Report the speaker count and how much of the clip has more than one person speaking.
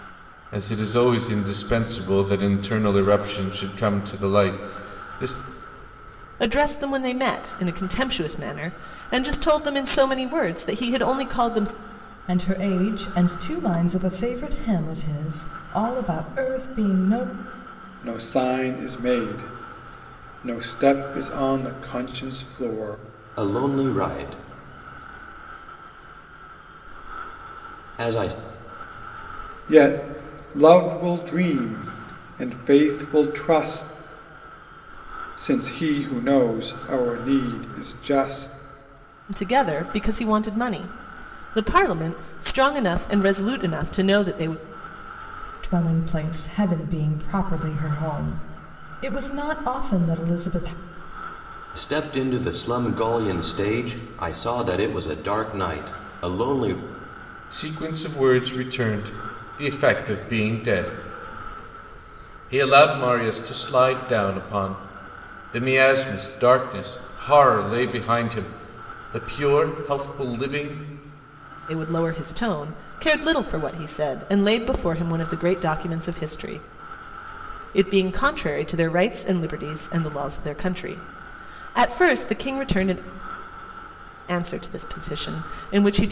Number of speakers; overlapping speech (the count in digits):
5, no overlap